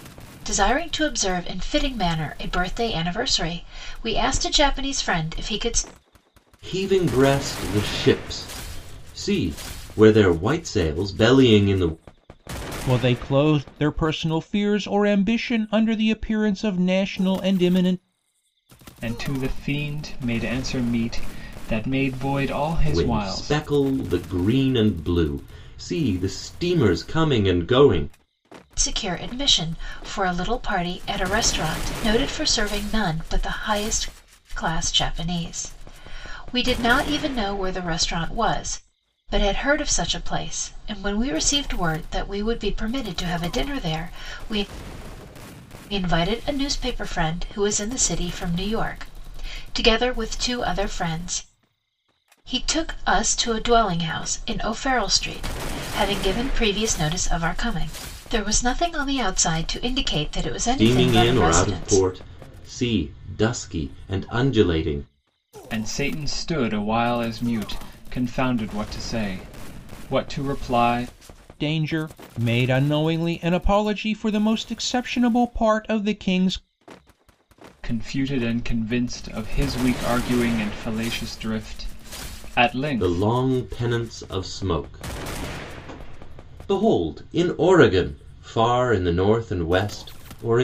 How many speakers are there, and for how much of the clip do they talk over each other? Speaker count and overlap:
4, about 3%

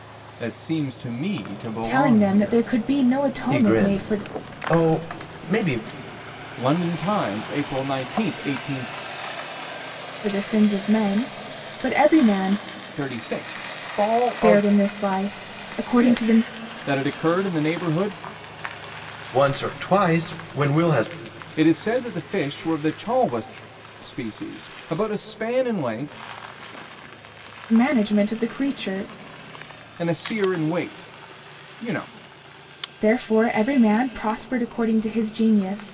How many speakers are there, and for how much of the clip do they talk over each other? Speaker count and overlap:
3, about 7%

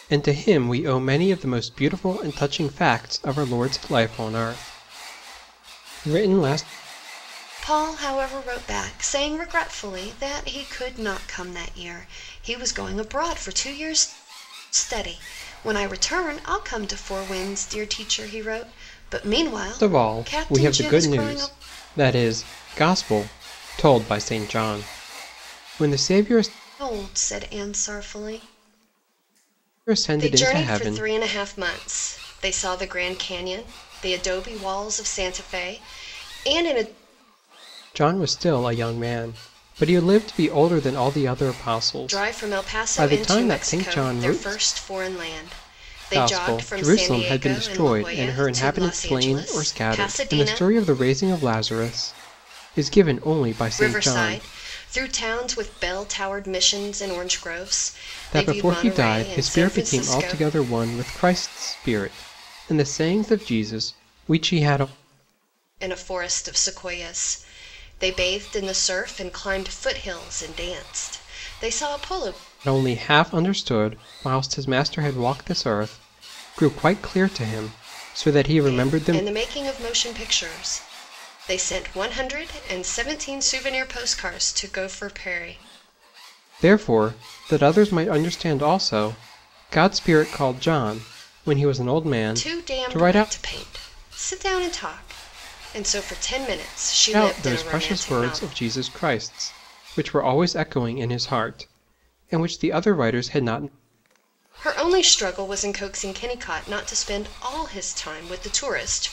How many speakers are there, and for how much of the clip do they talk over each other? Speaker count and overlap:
2, about 15%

